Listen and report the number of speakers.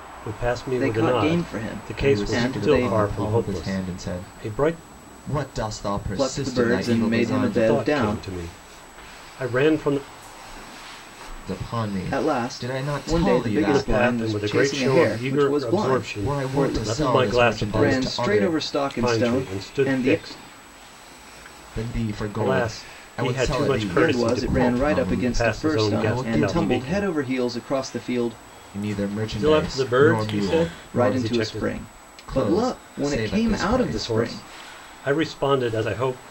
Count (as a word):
three